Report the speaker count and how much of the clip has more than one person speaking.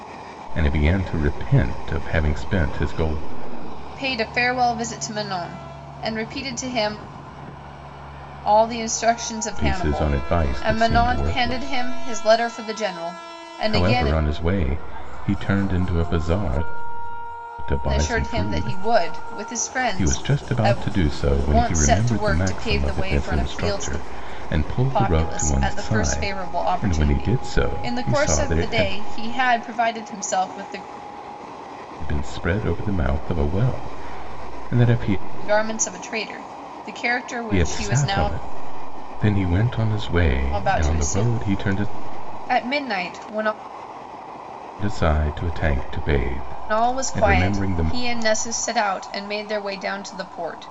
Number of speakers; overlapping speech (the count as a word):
two, about 28%